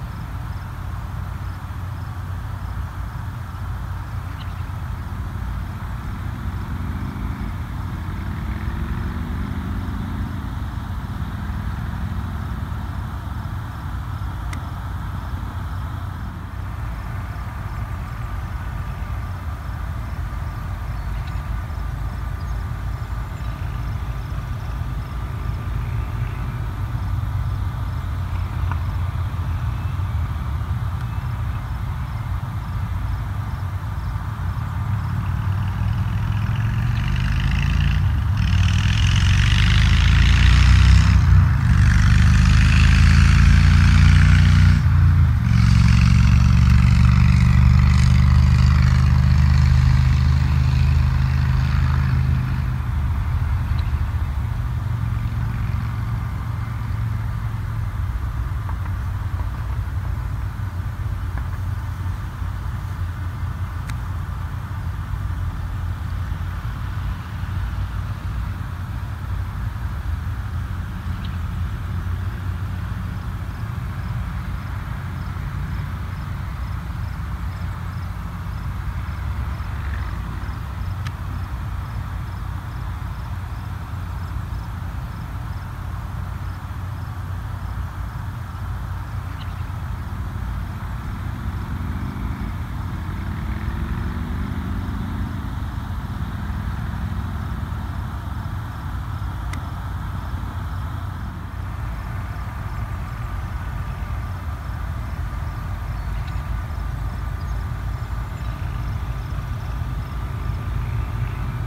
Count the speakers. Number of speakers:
0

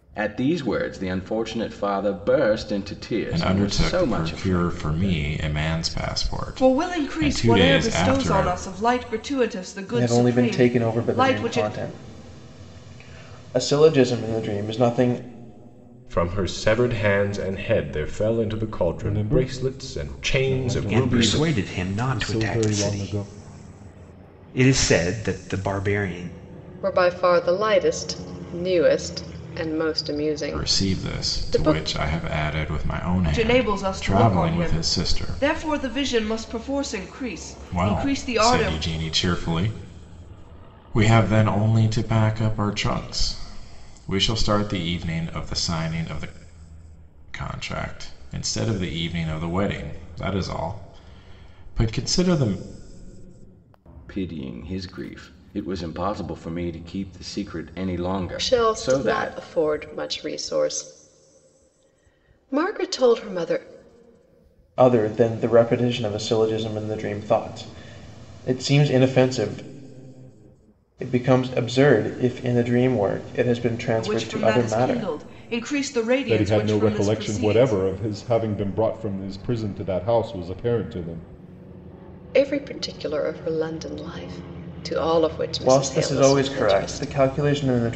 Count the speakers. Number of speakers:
8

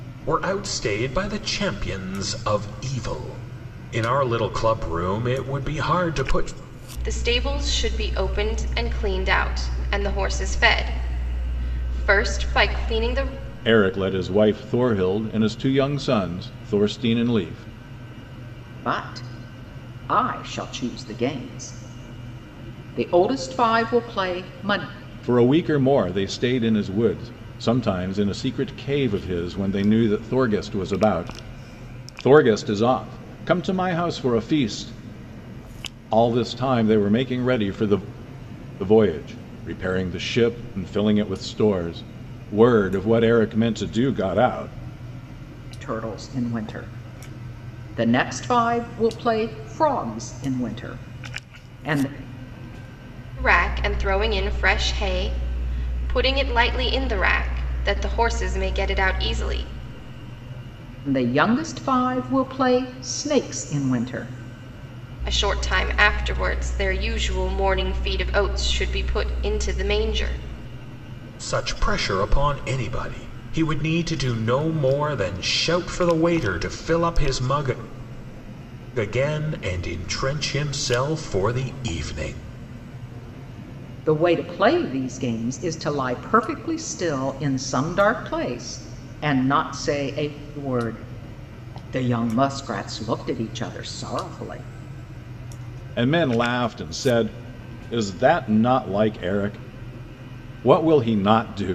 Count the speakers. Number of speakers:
4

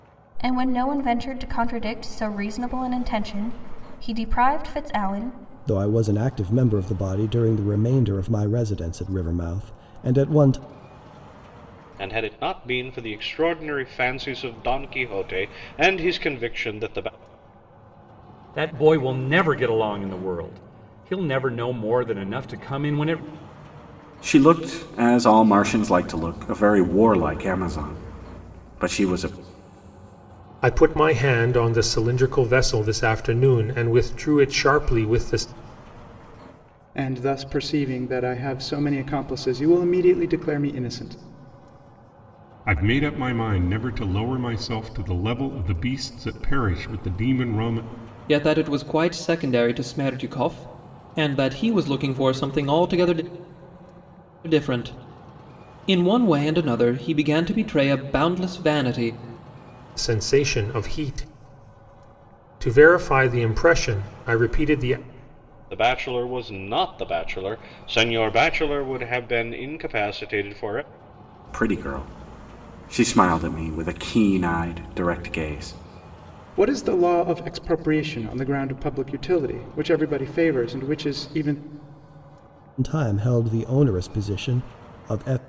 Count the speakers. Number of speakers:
9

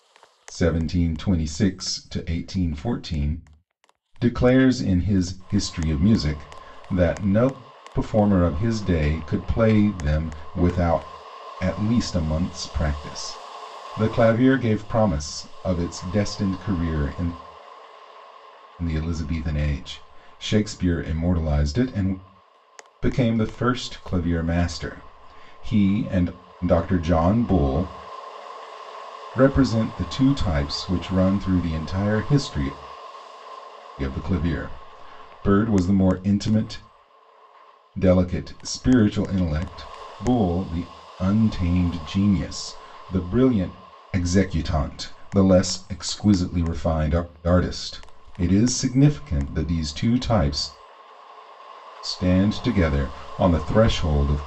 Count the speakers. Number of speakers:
1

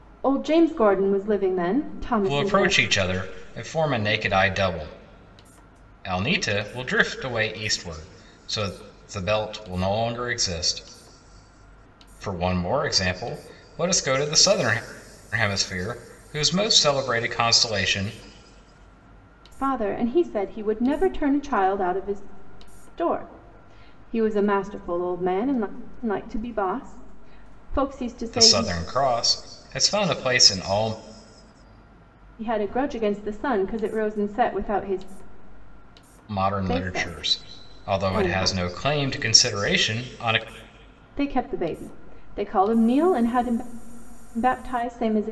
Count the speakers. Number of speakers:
2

